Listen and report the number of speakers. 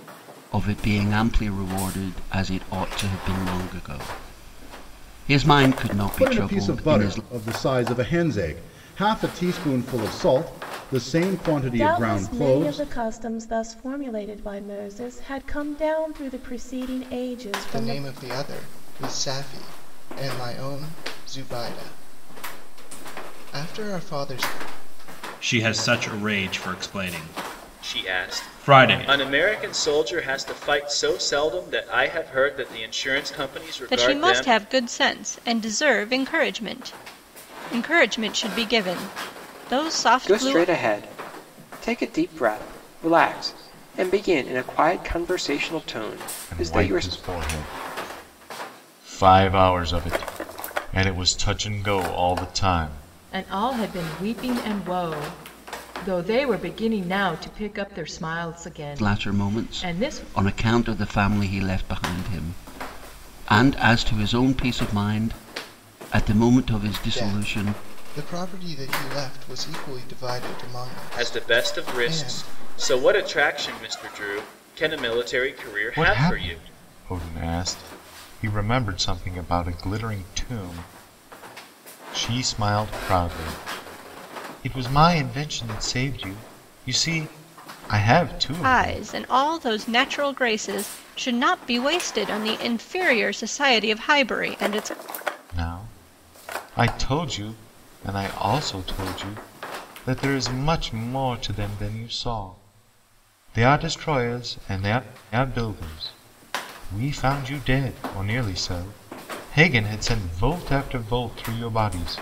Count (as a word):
ten